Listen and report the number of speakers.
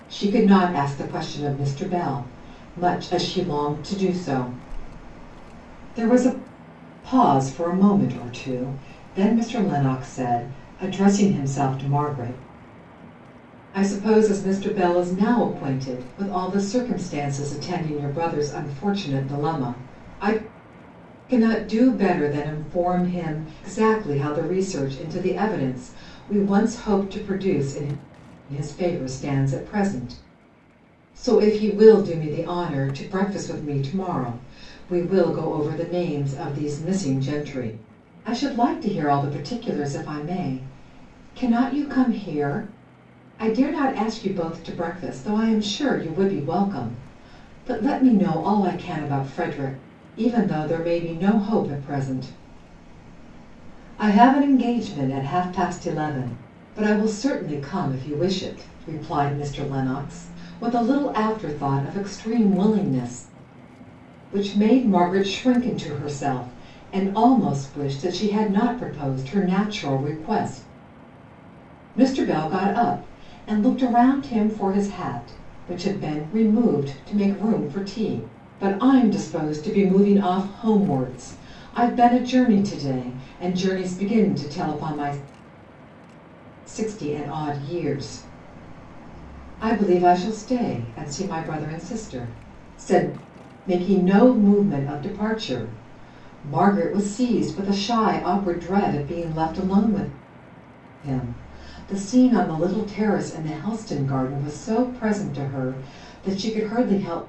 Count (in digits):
1